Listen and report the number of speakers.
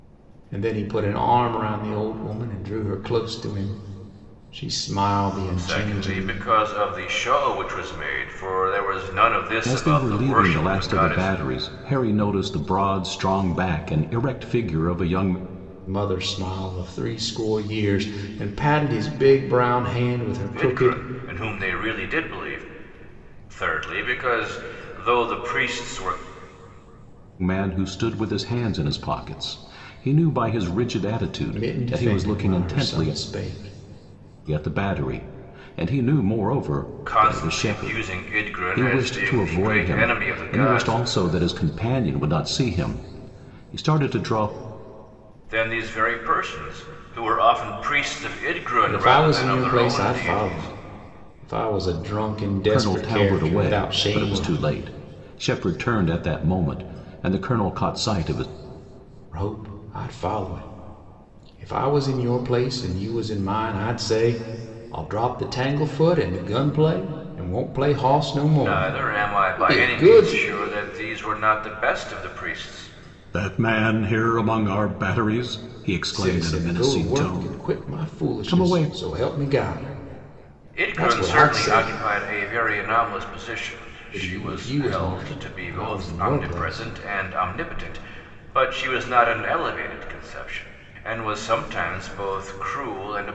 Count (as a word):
three